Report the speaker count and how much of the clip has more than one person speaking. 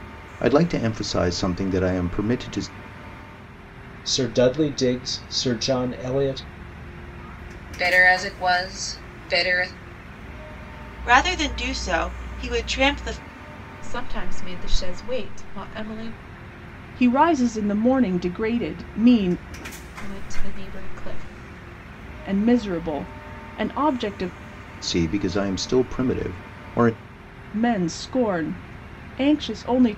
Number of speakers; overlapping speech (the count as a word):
six, no overlap